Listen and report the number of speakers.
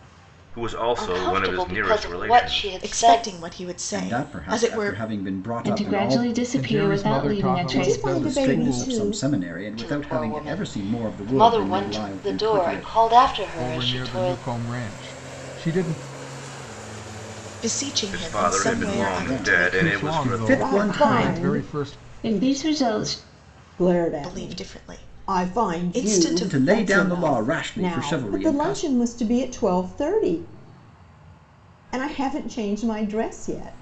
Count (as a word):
seven